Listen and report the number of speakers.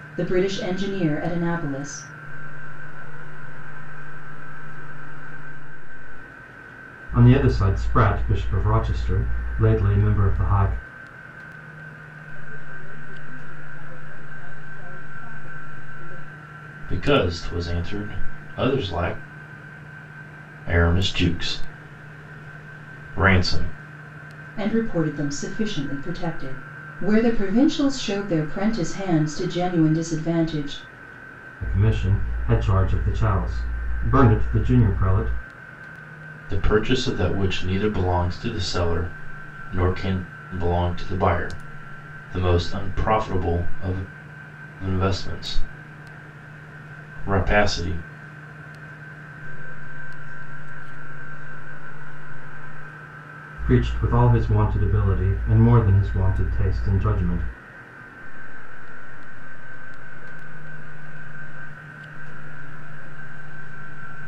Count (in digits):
5